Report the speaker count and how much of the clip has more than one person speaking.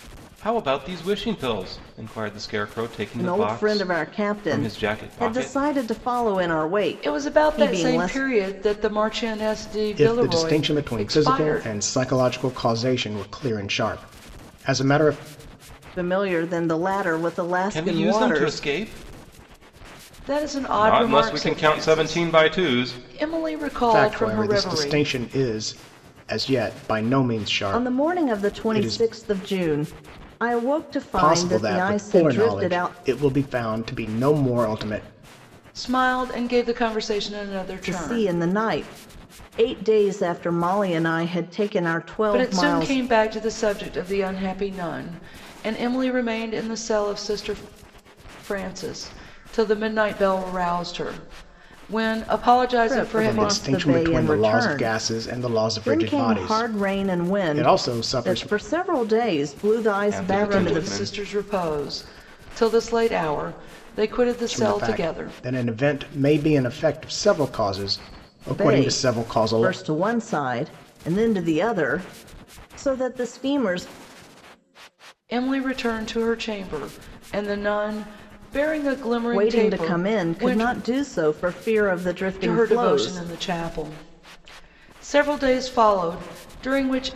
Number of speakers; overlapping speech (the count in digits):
4, about 29%